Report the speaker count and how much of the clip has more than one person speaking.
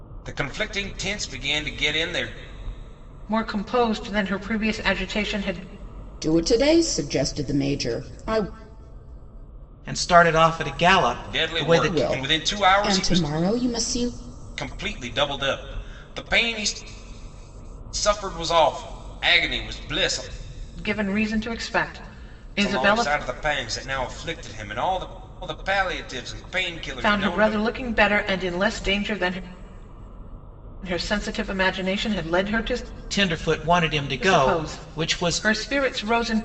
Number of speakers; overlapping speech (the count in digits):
4, about 12%